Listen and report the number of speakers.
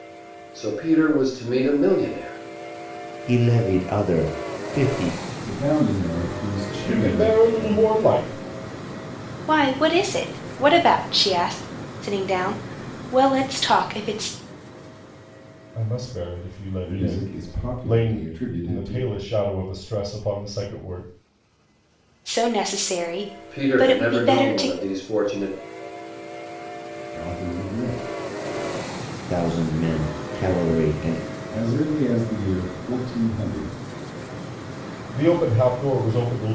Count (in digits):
5